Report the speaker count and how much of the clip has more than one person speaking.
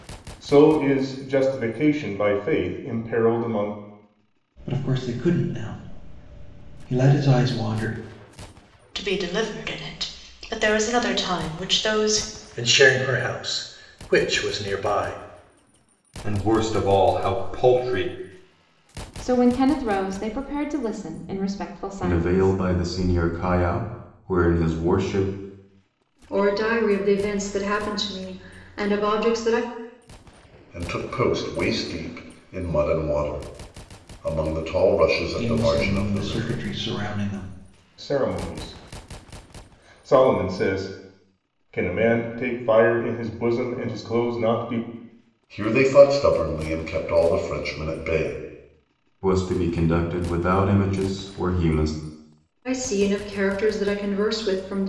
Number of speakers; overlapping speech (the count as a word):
nine, about 4%